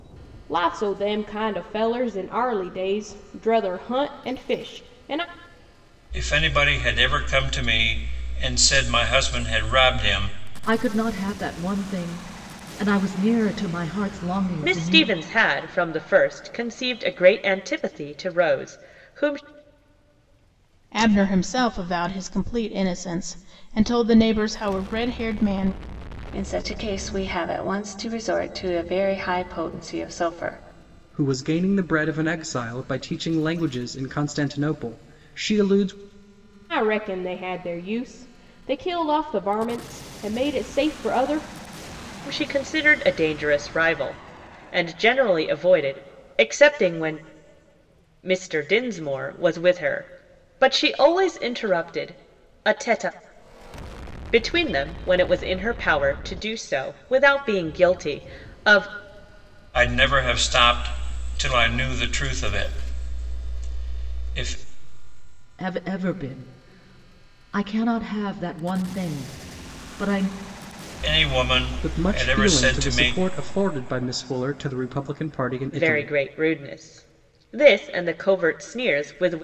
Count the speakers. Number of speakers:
7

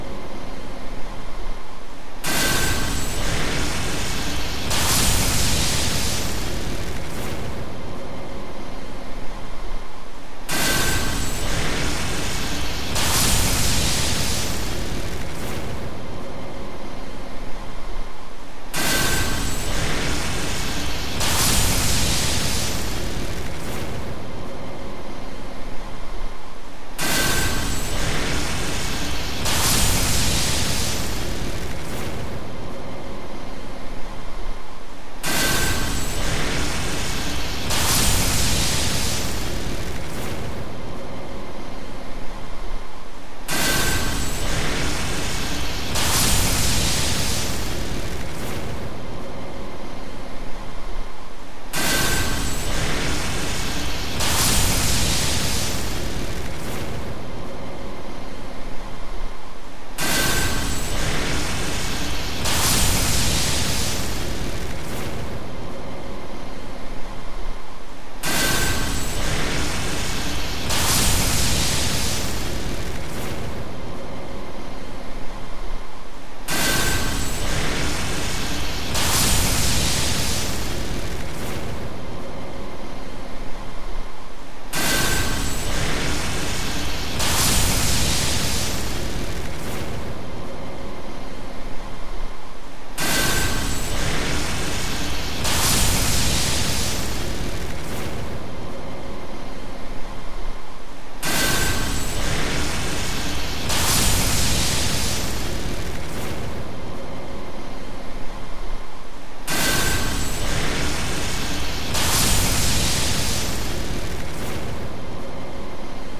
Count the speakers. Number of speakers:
0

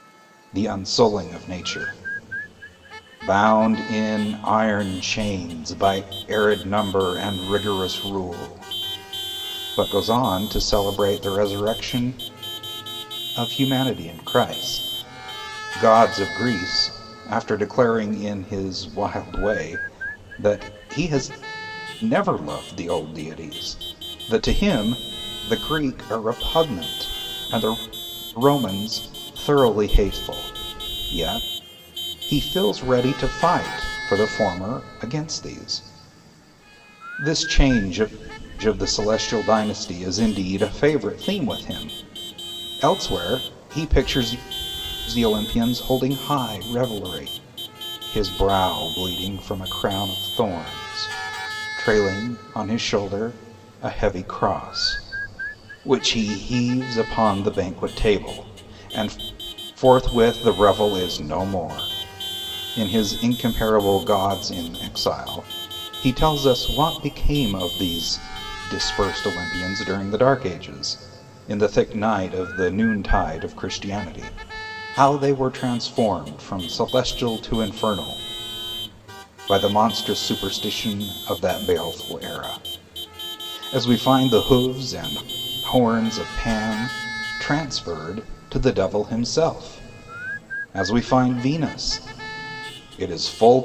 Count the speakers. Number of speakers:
1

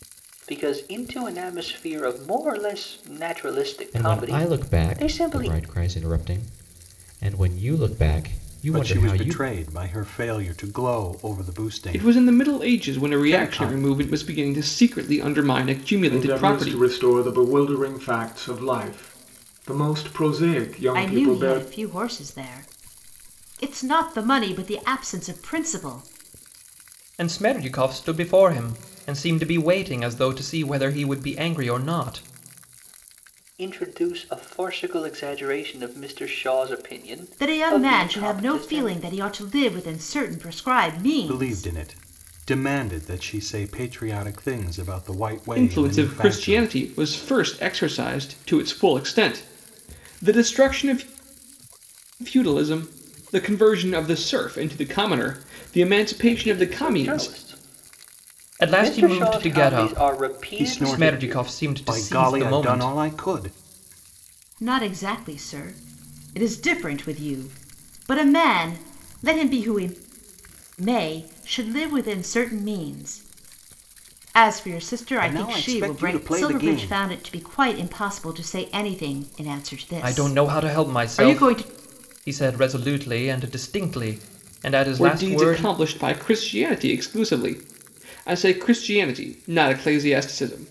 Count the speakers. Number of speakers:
7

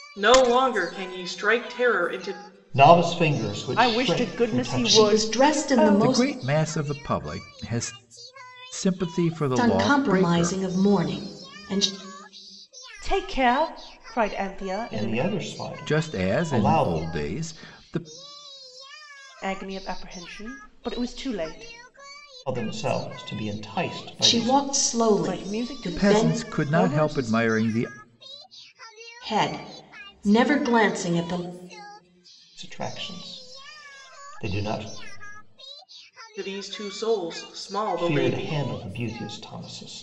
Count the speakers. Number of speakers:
5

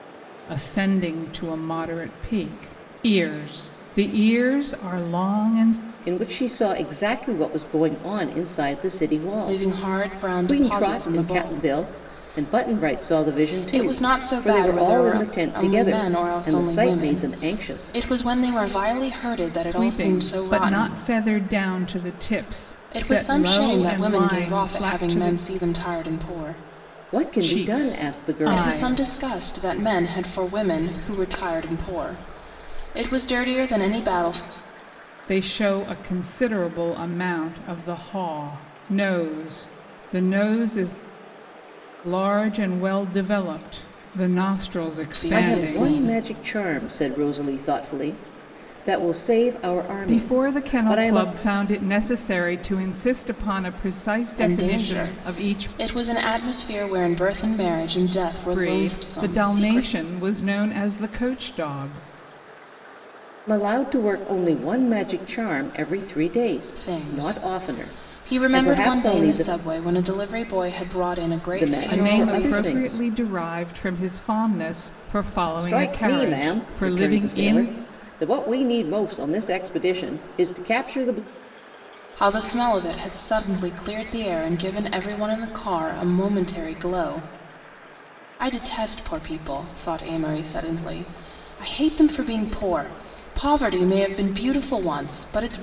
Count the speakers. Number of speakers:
3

